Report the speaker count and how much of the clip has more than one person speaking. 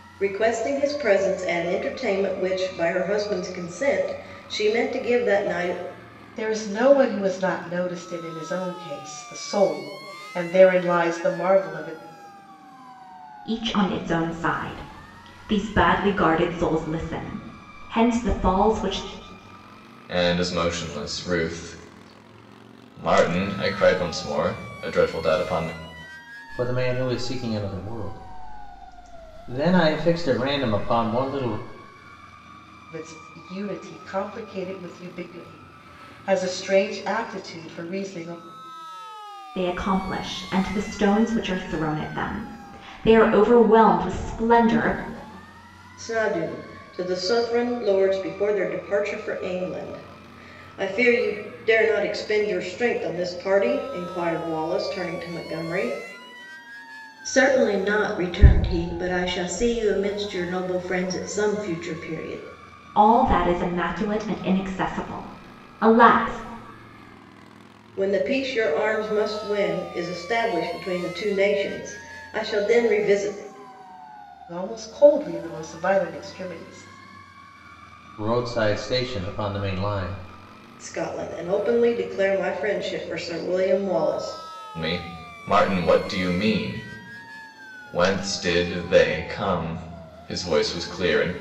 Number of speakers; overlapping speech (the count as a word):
five, no overlap